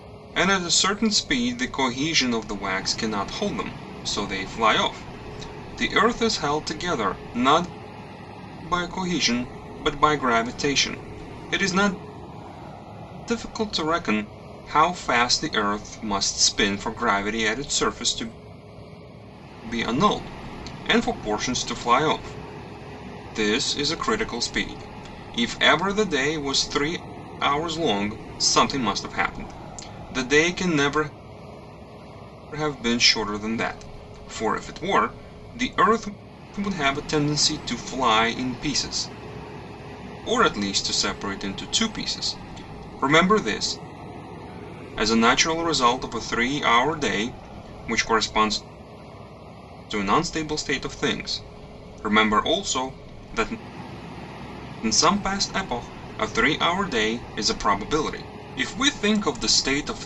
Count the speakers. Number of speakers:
1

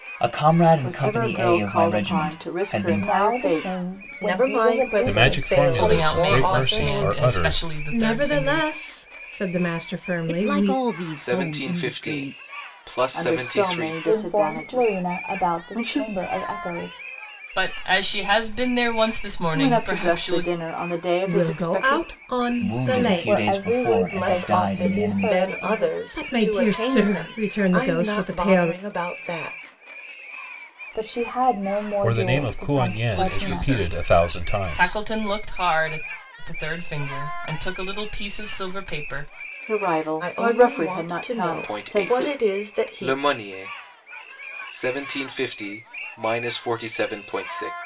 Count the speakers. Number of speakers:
9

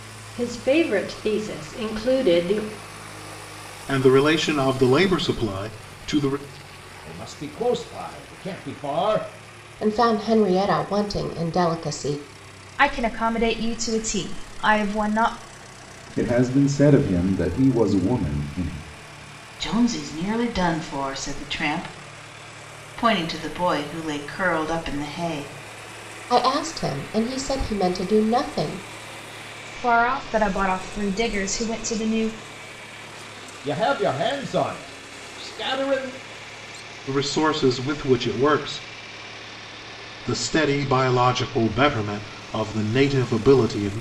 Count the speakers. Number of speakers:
7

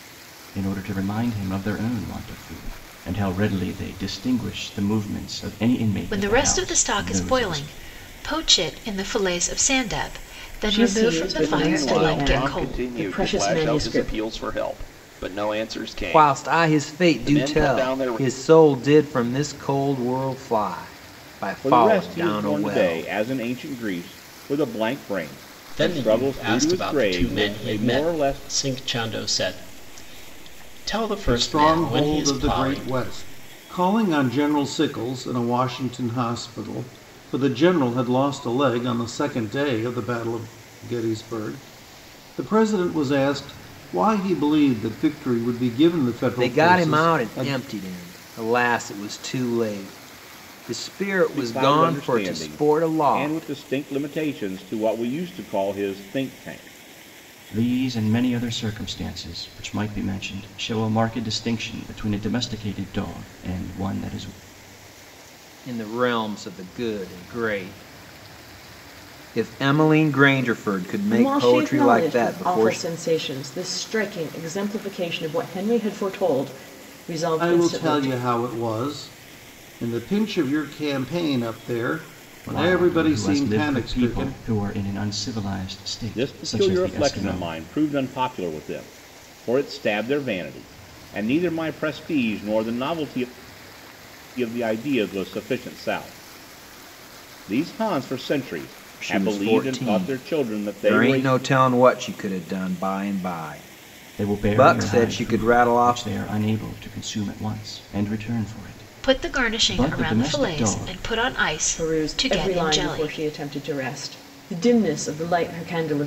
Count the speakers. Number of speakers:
8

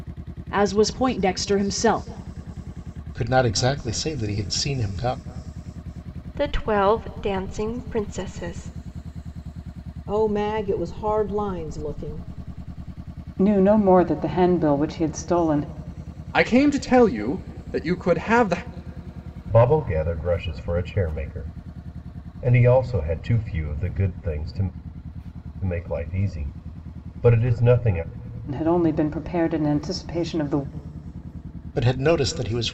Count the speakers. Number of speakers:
7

